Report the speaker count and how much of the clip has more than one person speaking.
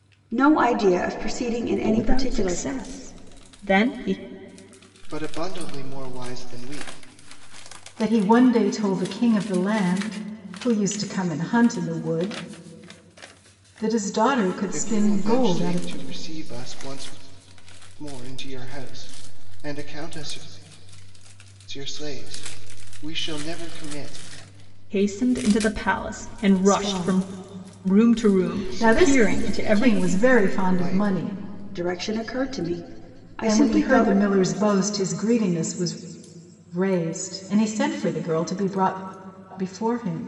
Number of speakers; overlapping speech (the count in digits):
4, about 16%